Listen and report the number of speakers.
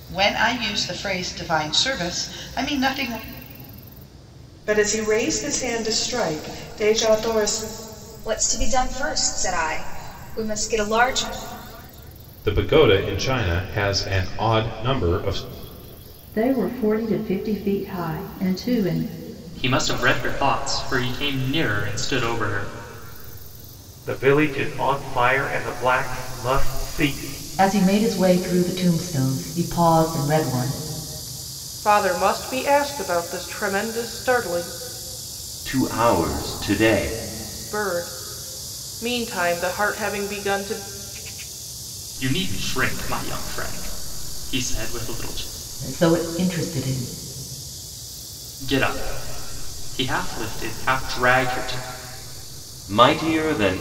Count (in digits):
10